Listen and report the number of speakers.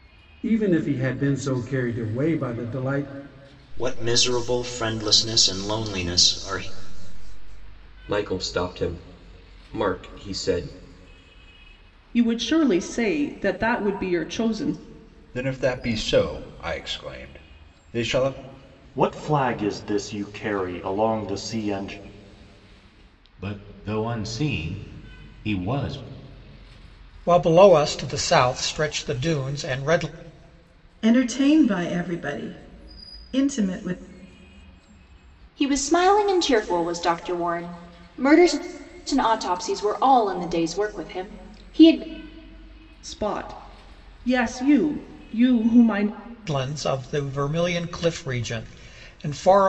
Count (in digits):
10